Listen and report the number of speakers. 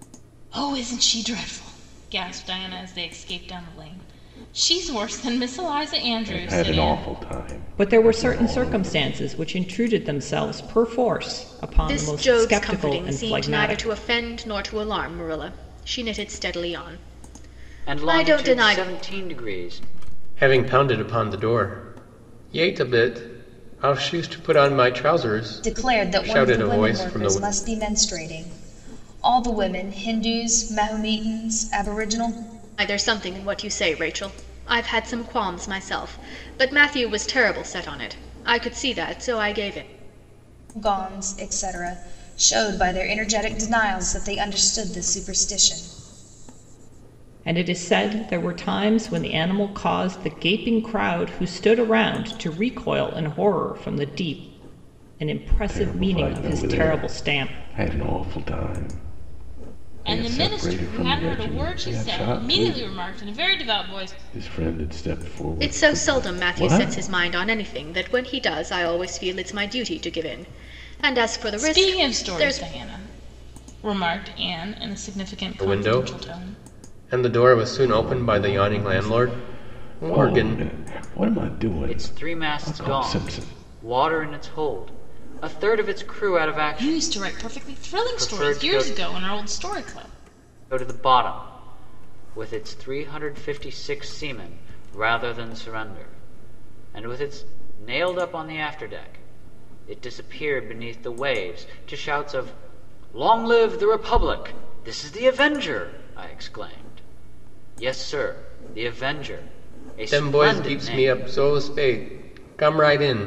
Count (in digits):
7